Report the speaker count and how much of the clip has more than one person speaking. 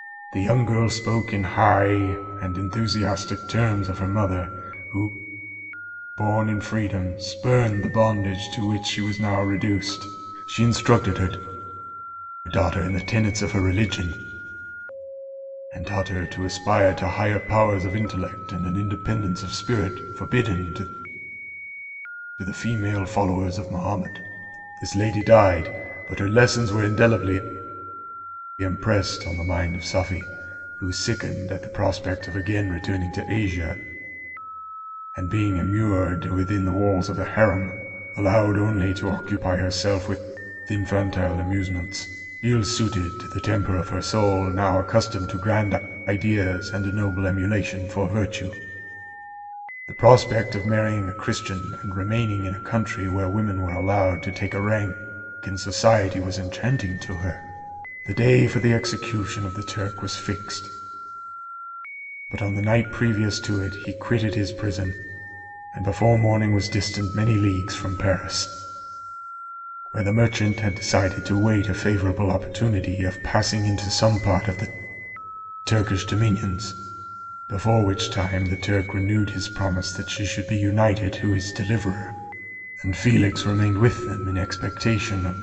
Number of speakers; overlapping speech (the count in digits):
1, no overlap